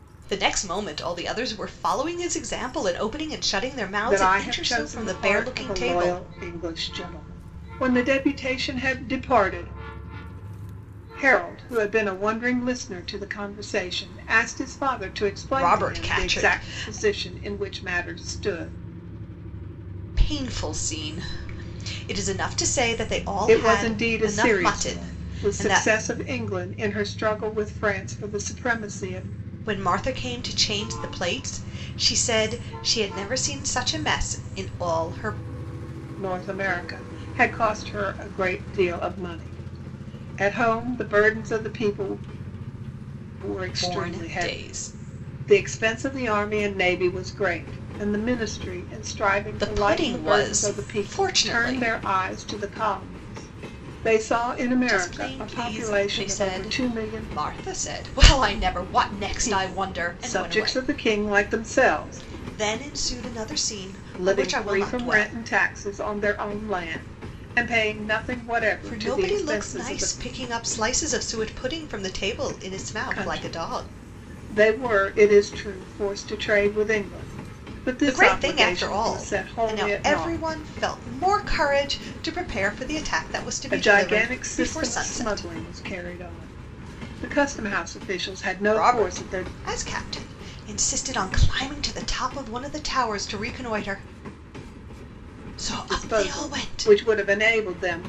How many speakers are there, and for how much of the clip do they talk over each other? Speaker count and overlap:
2, about 25%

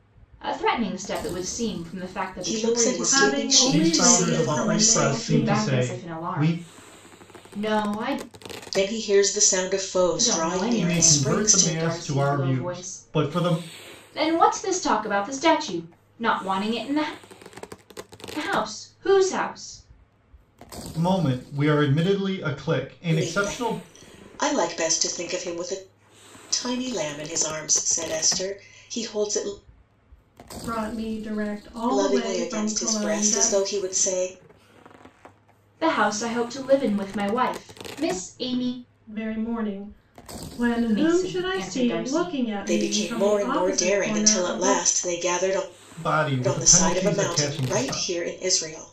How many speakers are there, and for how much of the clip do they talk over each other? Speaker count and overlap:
4, about 30%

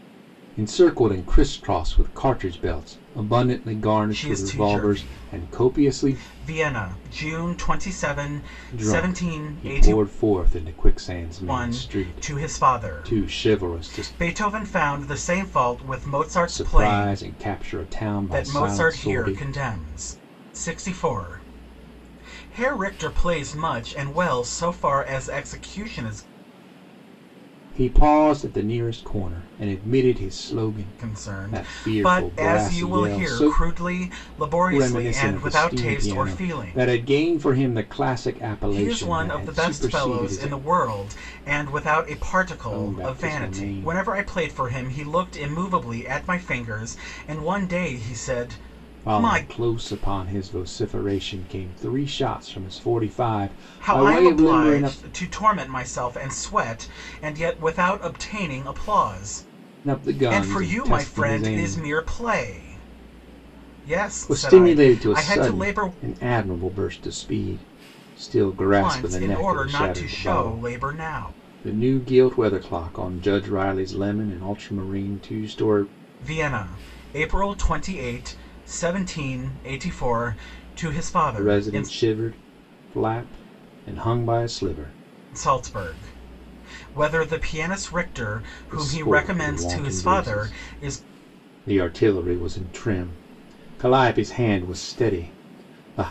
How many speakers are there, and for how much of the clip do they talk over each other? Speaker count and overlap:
2, about 28%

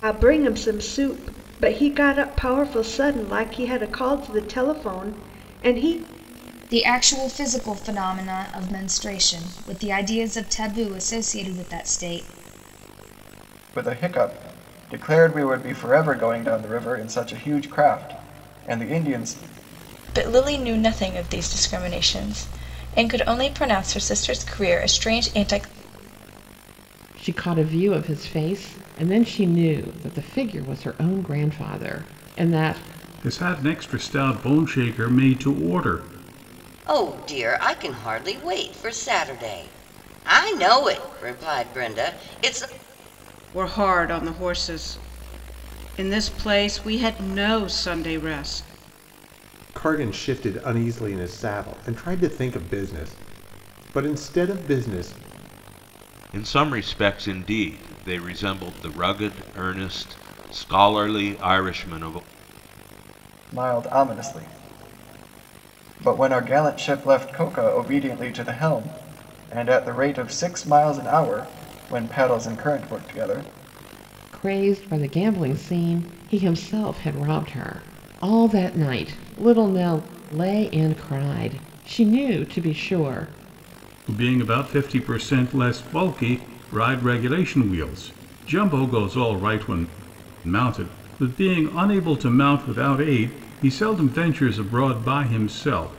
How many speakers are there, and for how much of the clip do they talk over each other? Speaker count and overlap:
10, no overlap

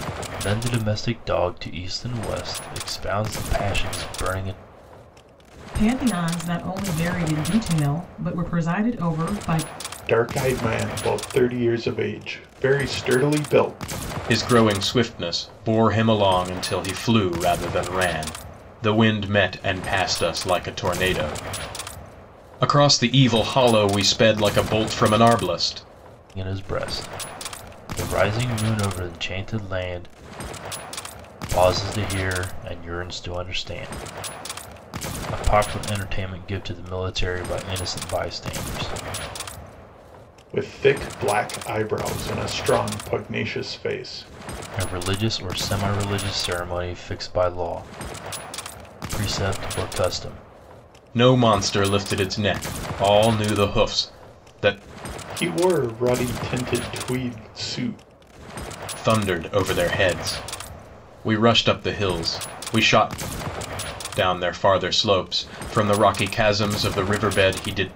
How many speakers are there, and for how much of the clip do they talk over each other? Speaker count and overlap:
4, no overlap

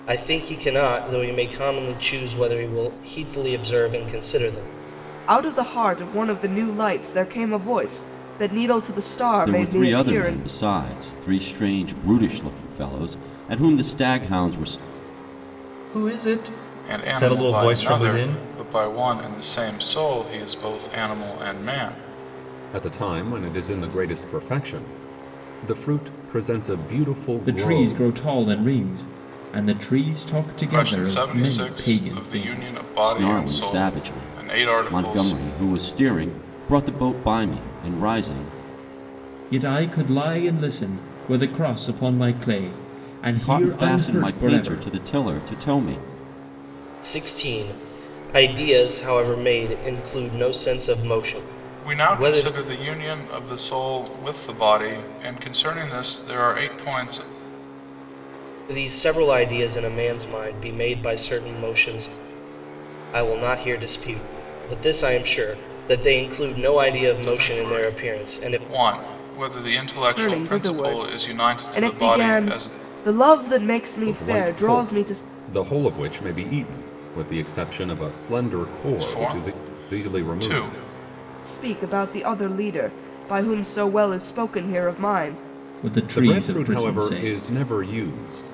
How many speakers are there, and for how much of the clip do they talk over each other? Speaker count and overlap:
7, about 21%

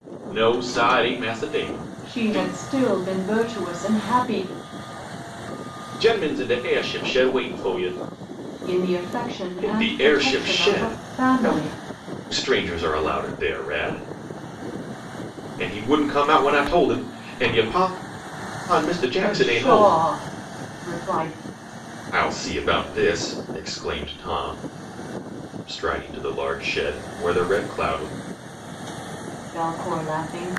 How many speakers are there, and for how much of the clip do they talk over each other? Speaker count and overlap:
2, about 11%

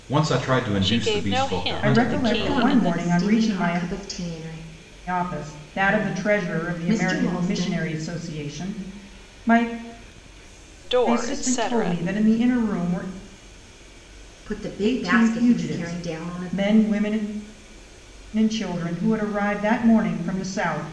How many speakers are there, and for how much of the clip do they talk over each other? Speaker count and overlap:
4, about 37%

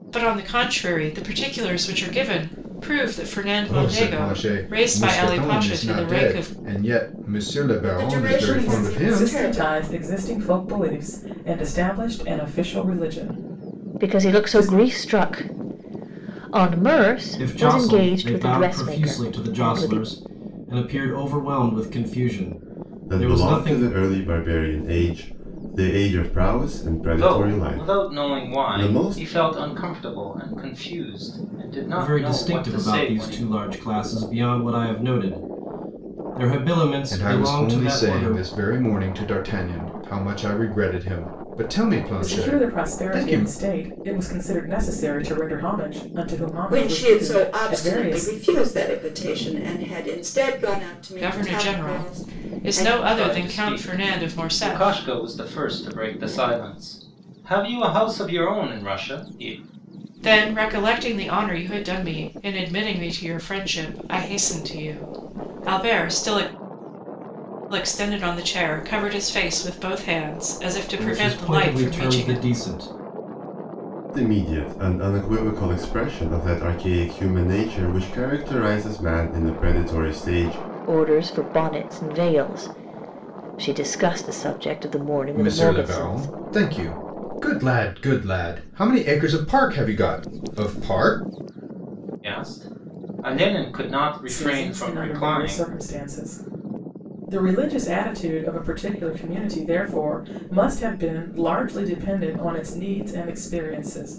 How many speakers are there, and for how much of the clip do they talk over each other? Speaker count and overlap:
8, about 24%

